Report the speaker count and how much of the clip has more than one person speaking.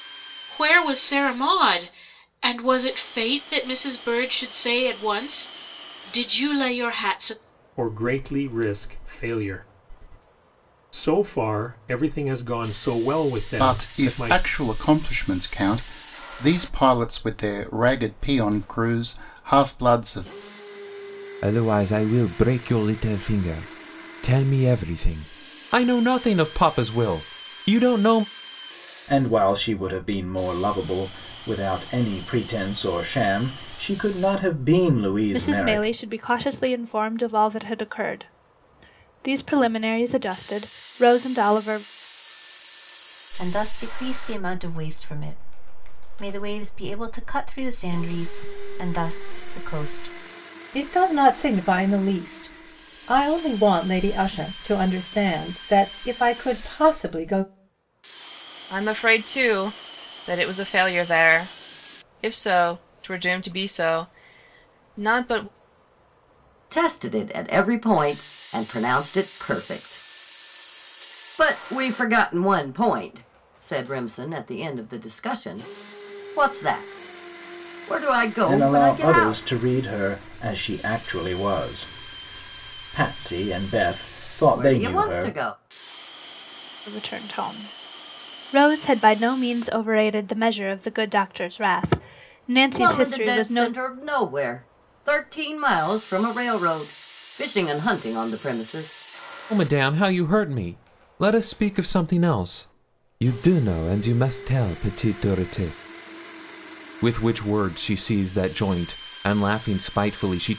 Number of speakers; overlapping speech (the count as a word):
ten, about 4%